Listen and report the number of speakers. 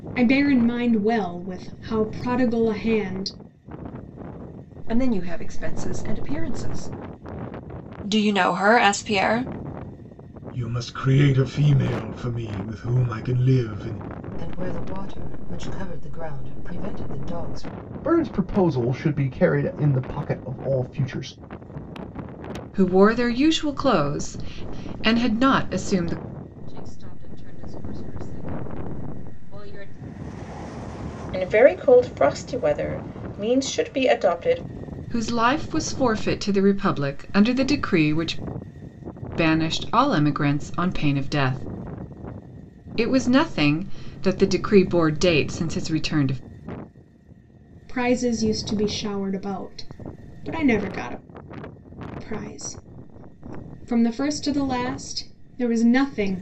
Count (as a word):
nine